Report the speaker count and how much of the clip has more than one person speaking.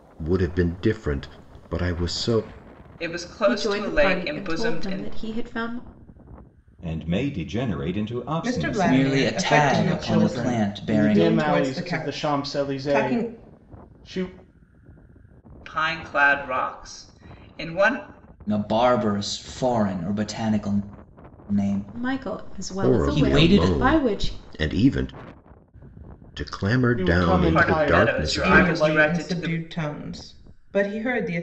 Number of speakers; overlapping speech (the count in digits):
7, about 37%